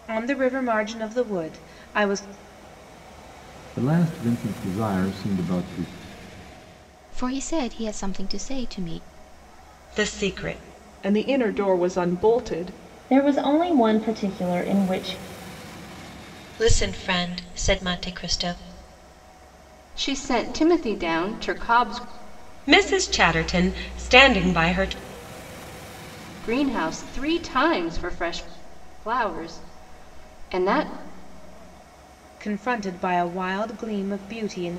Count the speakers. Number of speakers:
eight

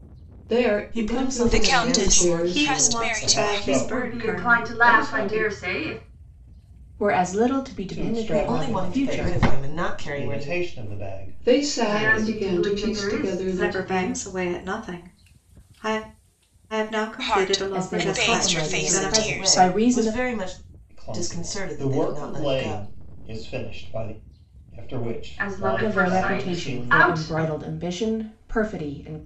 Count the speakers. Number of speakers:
seven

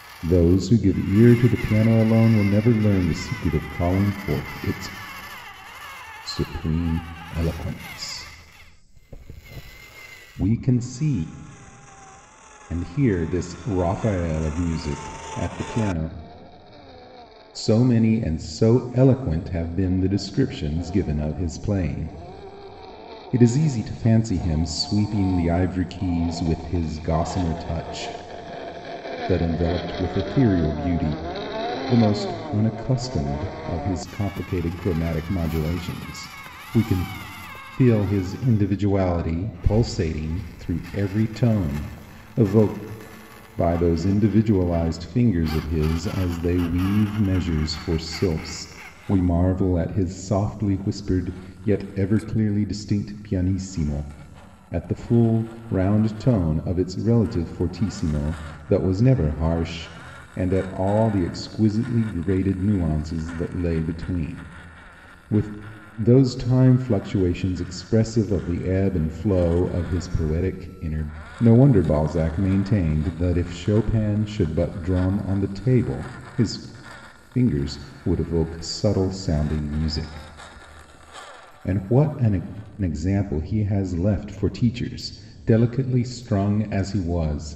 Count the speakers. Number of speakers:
one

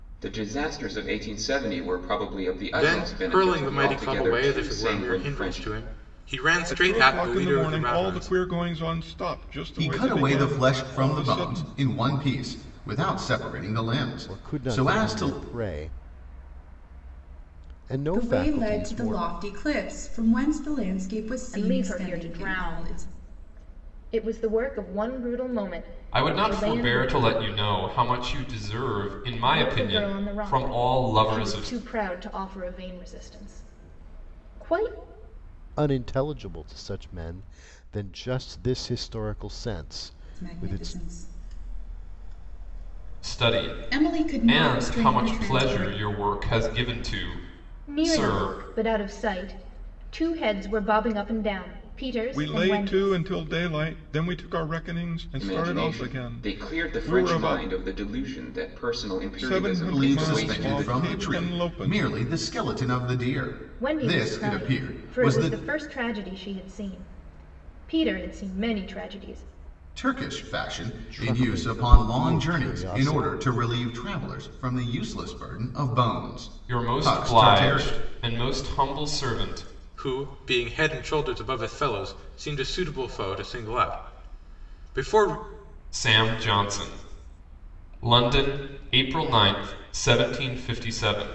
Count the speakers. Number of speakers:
eight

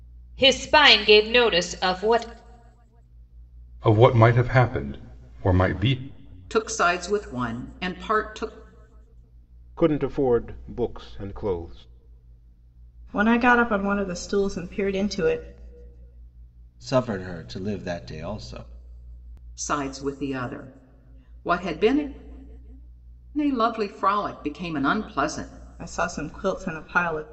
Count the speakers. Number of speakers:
six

